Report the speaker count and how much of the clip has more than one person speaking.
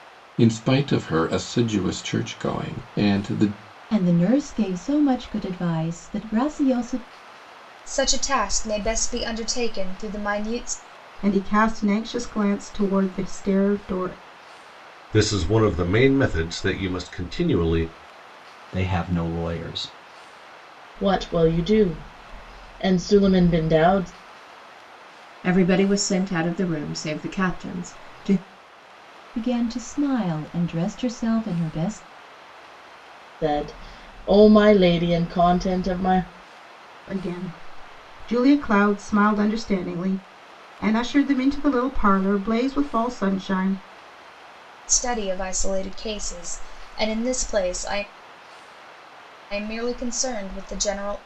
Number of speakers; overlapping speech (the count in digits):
8, no overlap